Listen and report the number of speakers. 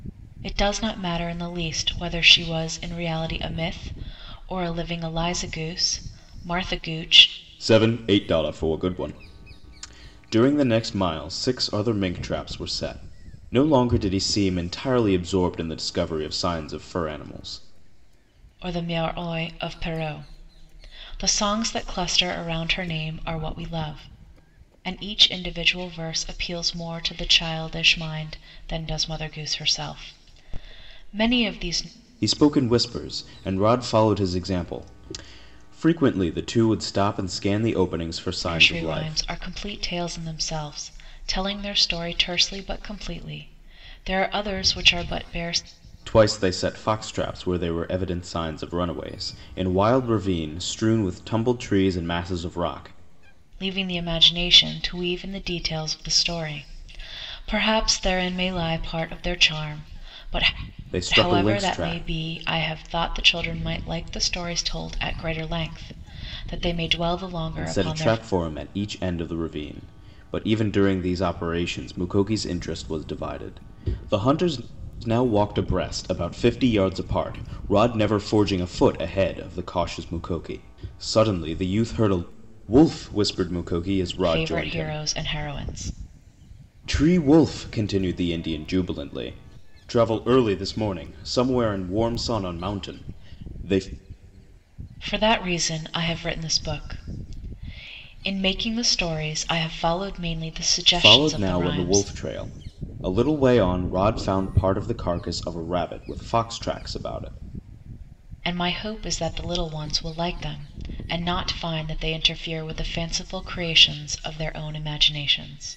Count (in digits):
2